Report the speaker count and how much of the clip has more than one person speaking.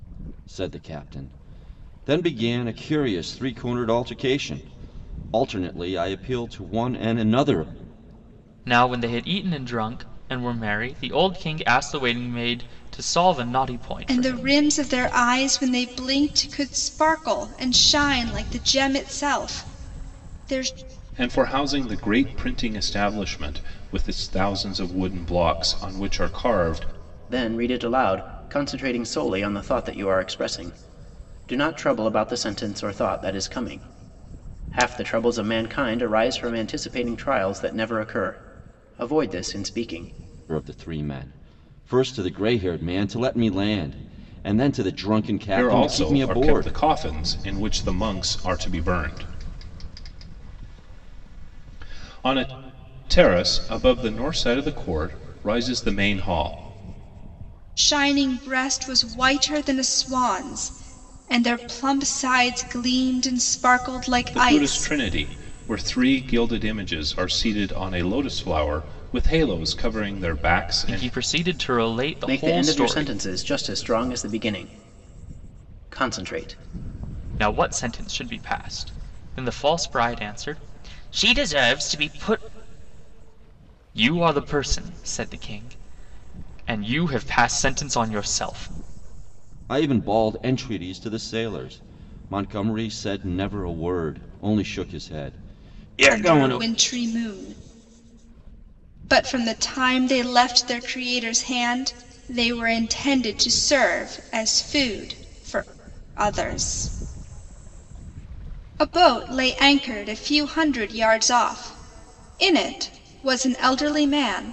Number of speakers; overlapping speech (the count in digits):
5, about 4%